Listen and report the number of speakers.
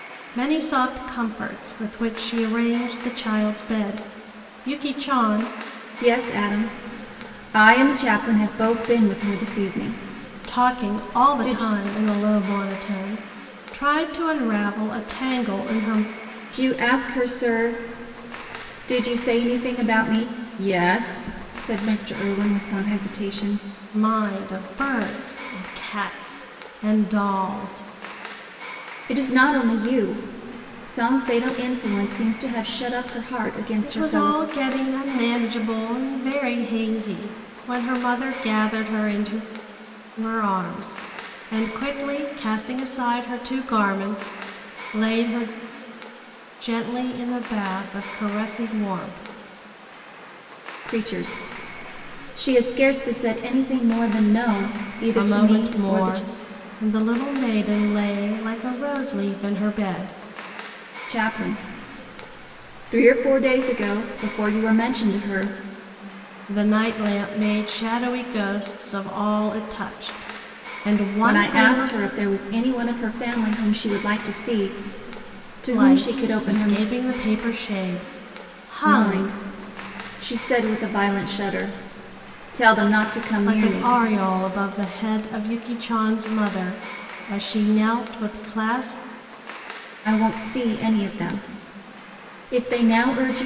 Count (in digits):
2